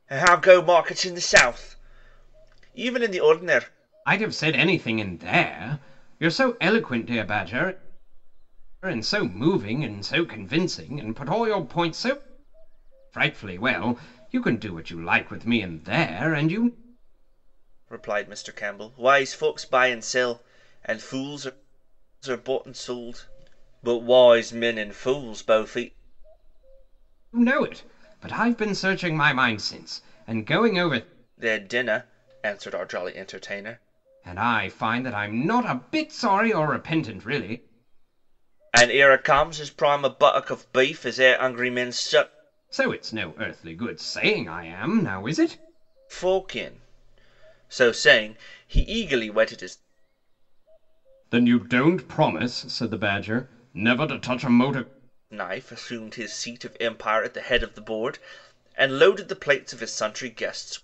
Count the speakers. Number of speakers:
two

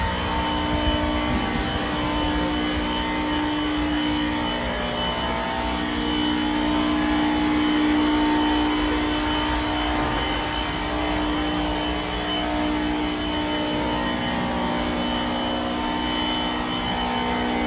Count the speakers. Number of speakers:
zero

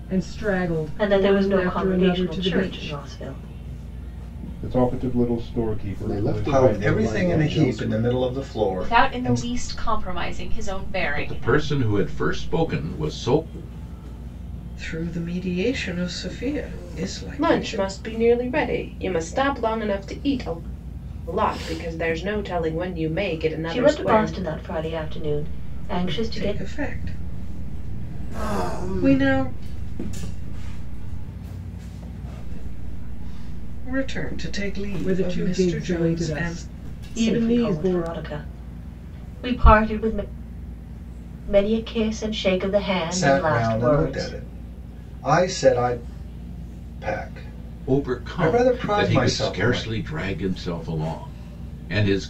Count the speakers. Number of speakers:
ten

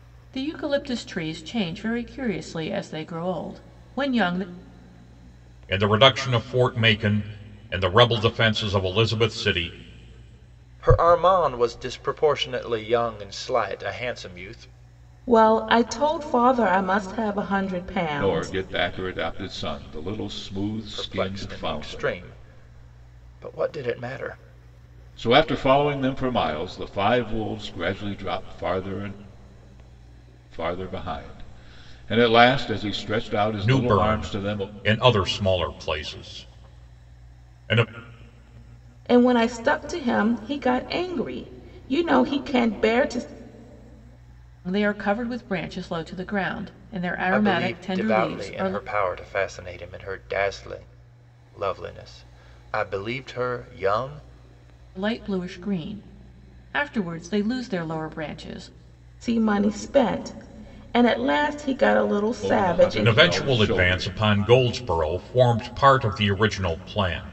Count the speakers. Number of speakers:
five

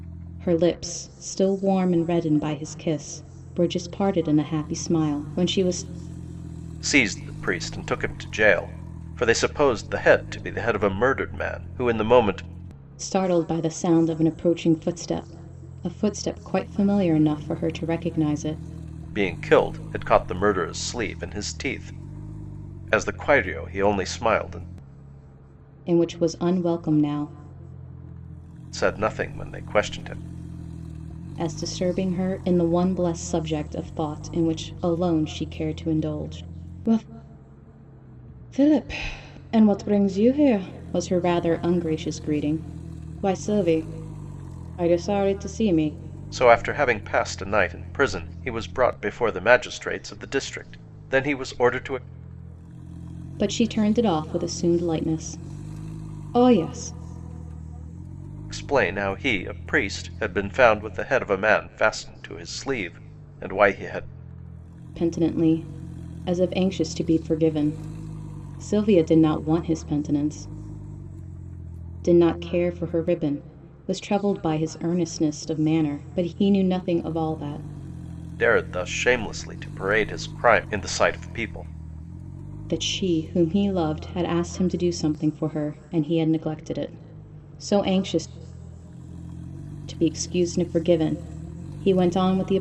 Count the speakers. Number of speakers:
two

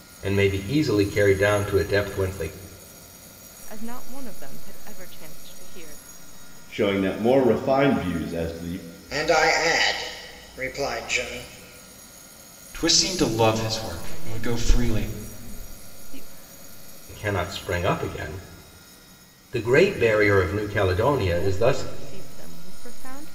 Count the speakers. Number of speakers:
five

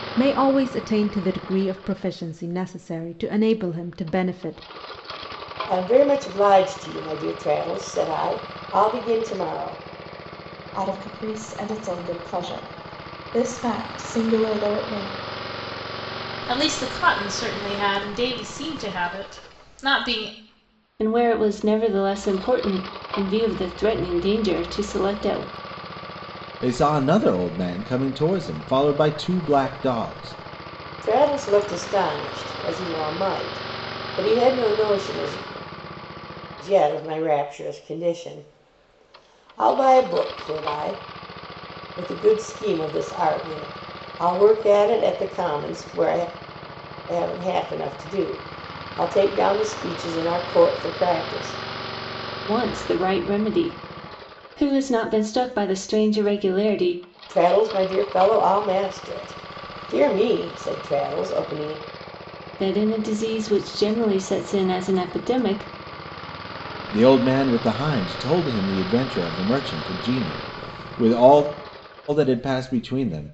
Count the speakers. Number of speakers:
six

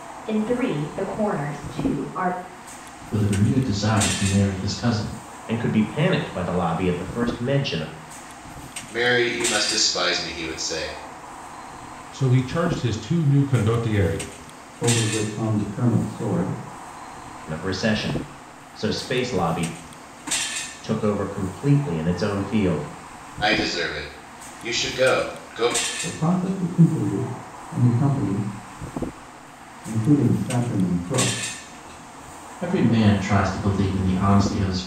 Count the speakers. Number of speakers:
six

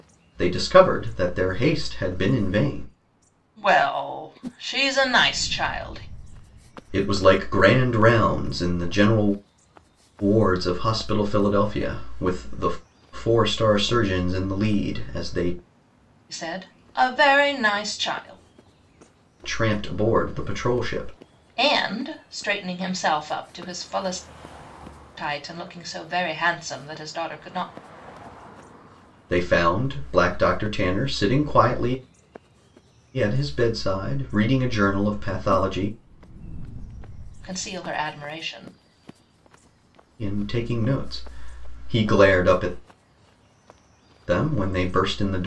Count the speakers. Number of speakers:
two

